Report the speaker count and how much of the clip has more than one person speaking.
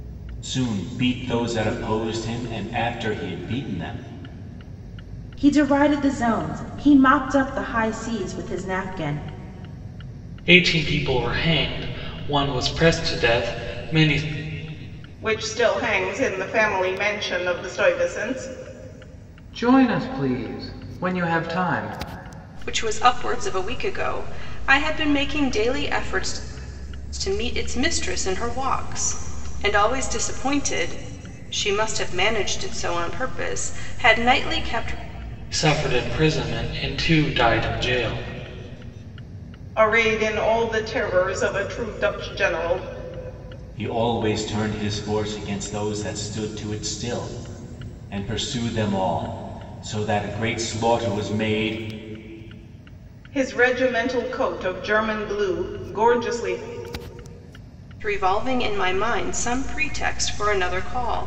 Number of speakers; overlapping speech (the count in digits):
6, no overlap